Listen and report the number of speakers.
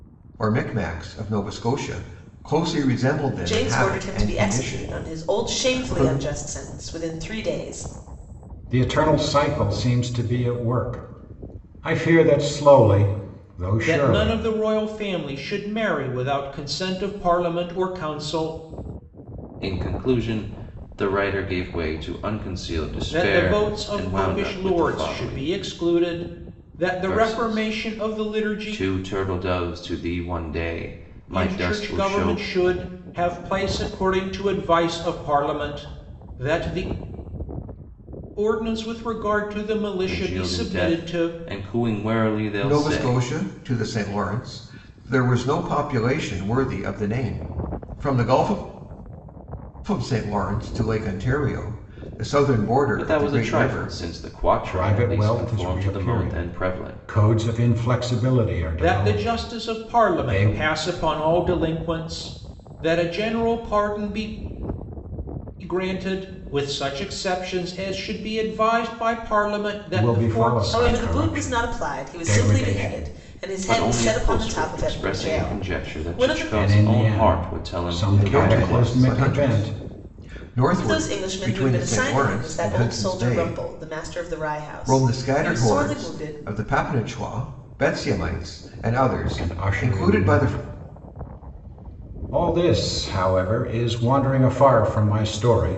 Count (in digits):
5